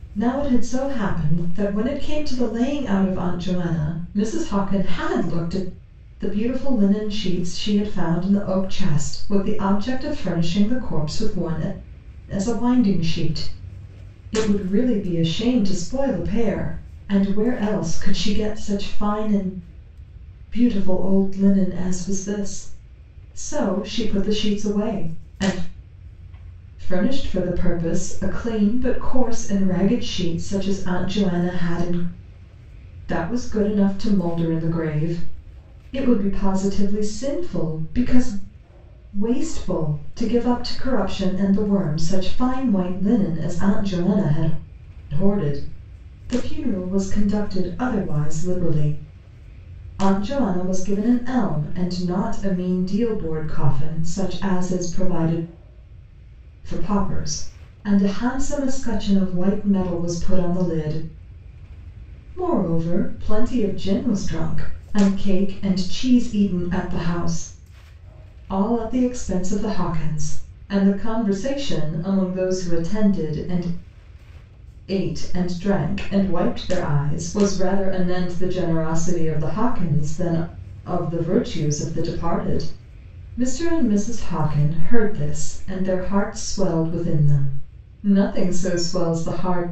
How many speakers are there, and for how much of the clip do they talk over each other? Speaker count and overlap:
1, no overlap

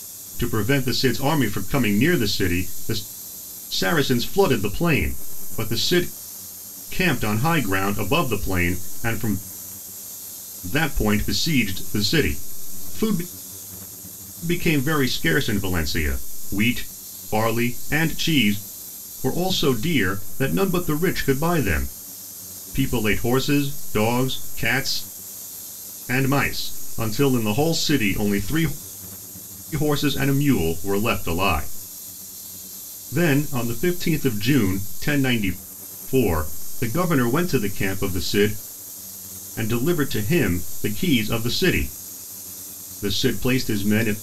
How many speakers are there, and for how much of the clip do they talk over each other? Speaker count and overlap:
1, no overlap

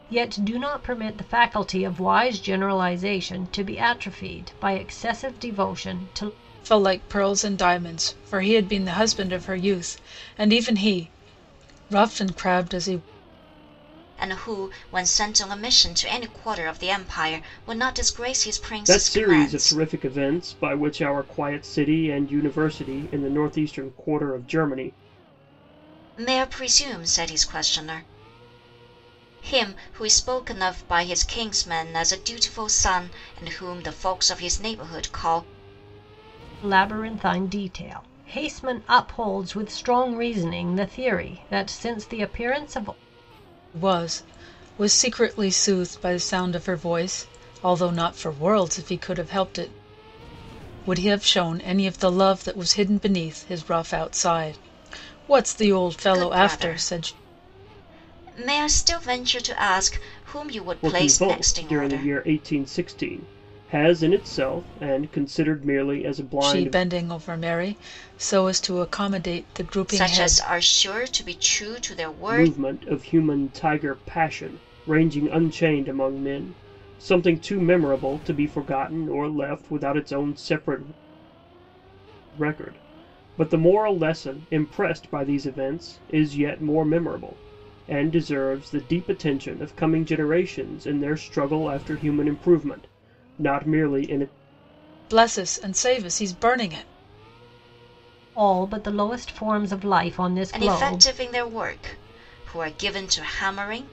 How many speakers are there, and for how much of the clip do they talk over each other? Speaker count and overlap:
4, about 5%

